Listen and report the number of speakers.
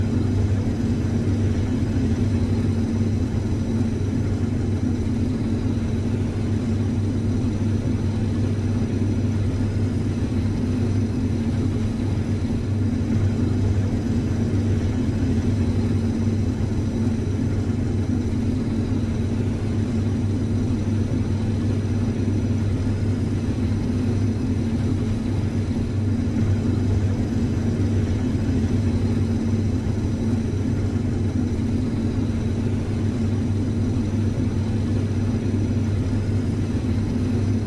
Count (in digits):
0